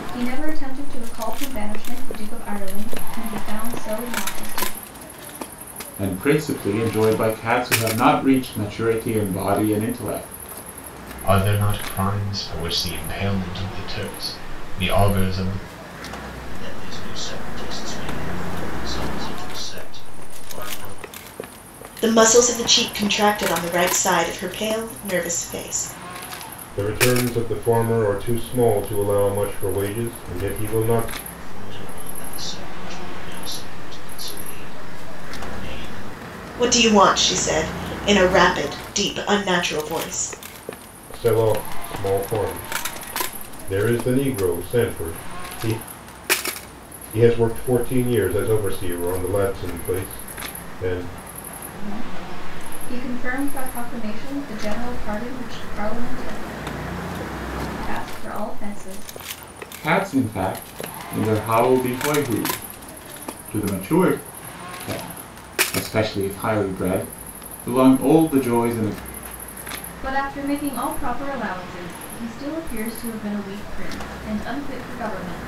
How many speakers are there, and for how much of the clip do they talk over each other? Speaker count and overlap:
6, no overlap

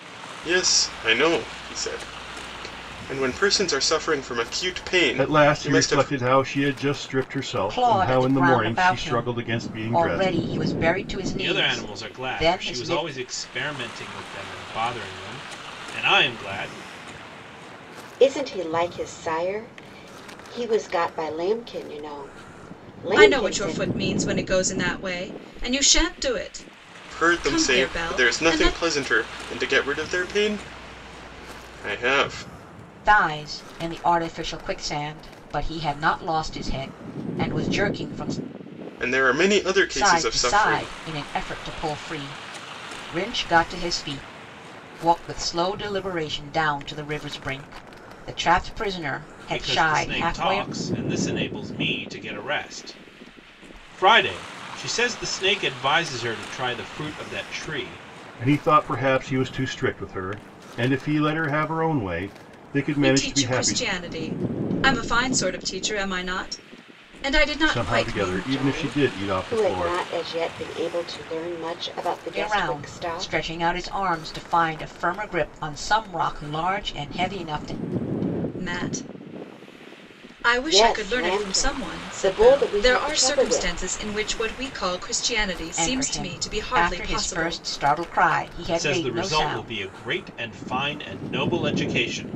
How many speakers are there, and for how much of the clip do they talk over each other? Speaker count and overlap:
6, about 23%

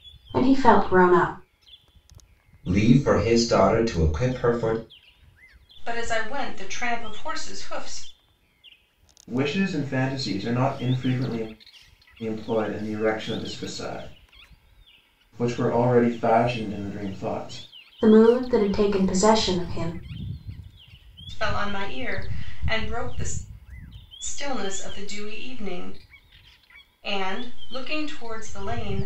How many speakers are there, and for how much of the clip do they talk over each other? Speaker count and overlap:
4, no overlap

